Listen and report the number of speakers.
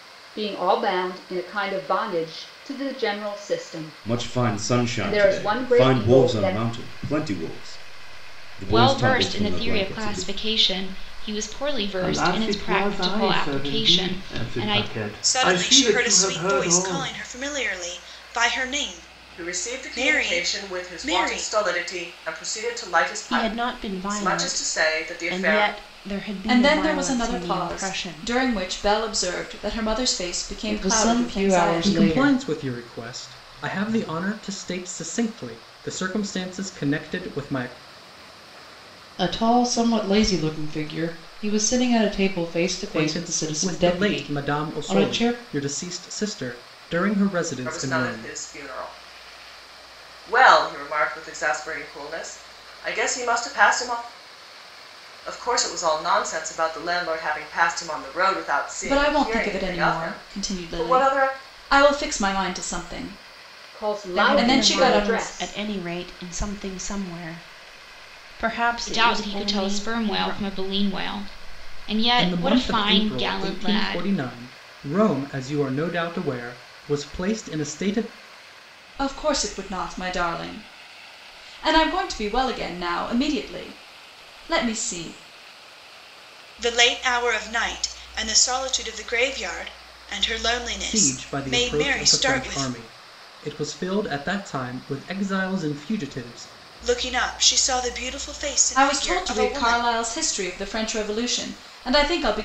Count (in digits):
10